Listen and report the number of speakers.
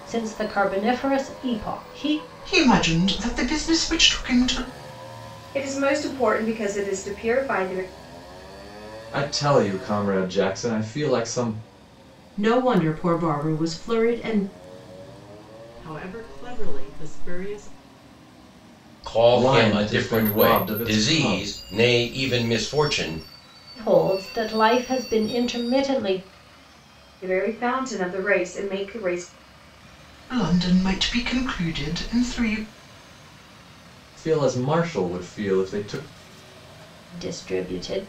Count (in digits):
7